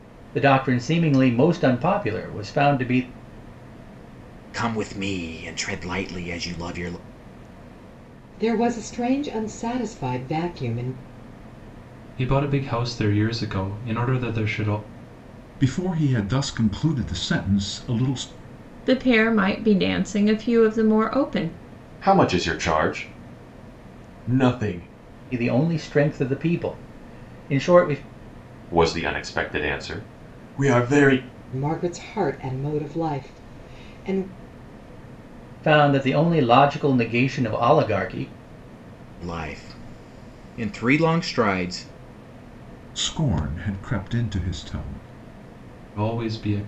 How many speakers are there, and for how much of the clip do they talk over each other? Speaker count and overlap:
7, no overlap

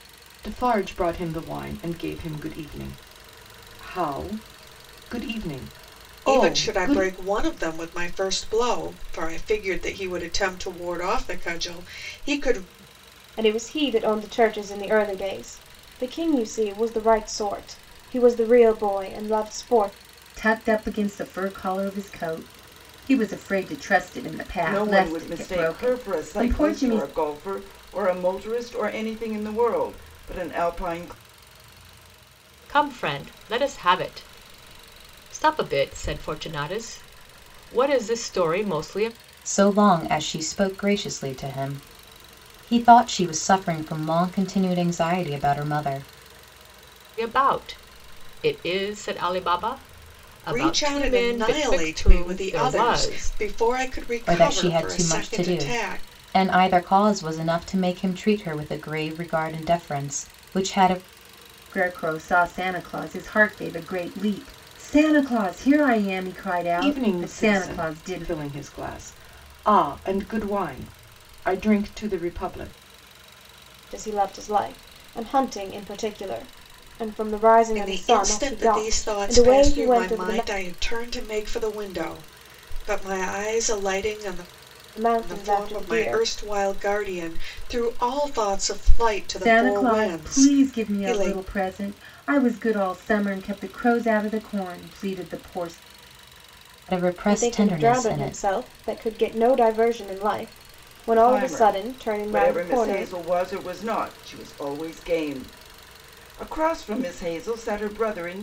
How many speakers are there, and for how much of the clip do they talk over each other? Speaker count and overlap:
7, about 17%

